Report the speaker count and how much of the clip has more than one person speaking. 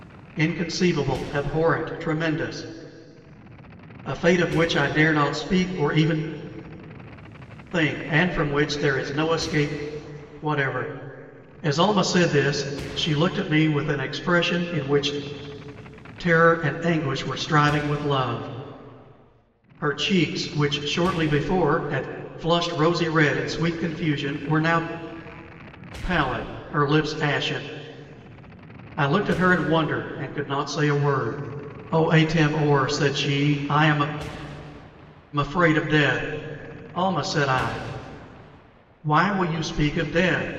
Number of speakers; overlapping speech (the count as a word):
one, no overlap